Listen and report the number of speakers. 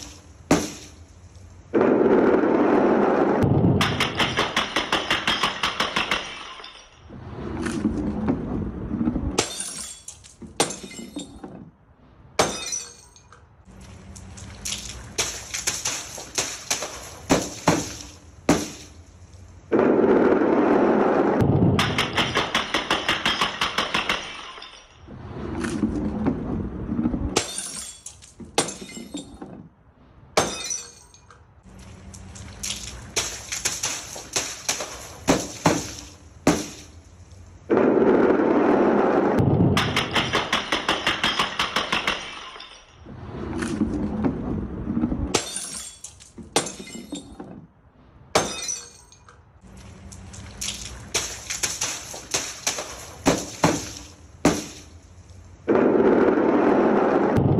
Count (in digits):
0